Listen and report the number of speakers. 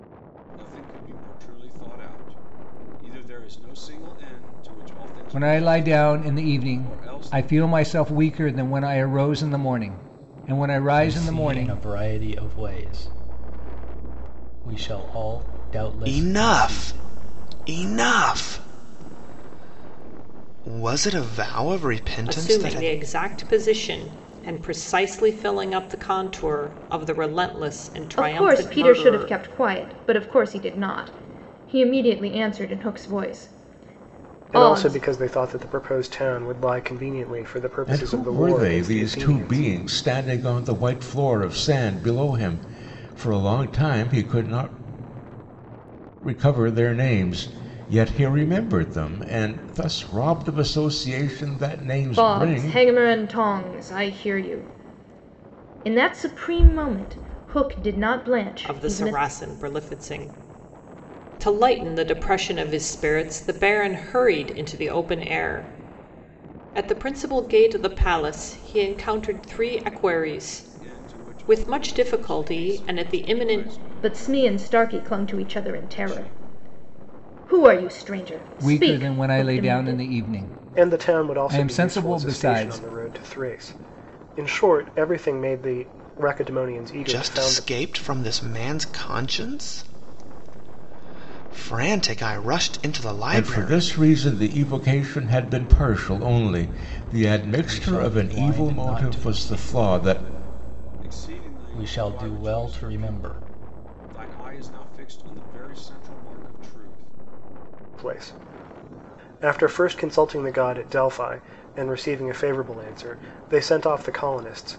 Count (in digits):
8